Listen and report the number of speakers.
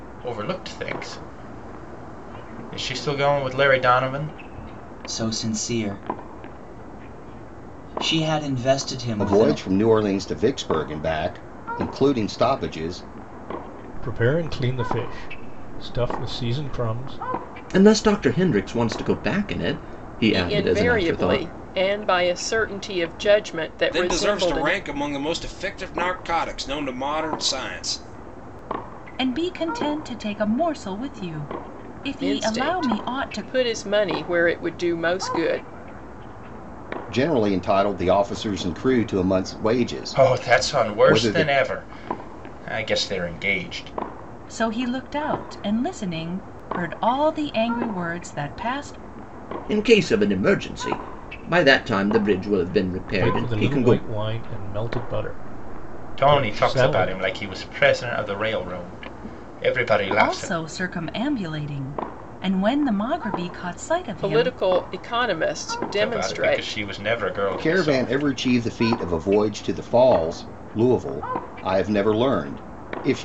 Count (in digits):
8